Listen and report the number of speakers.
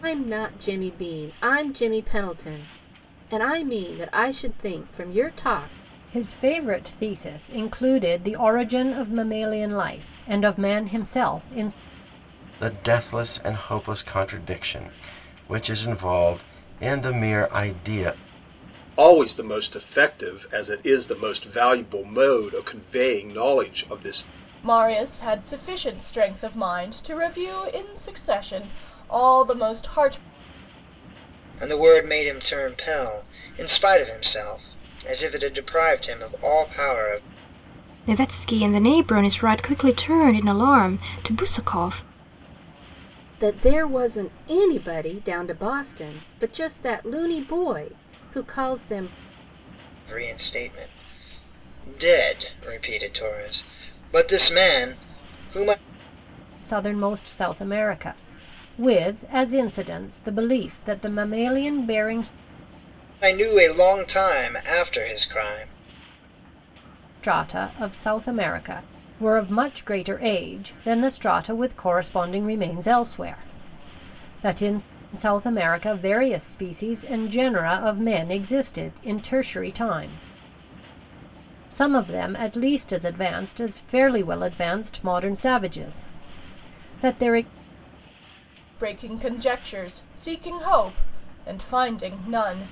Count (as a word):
seven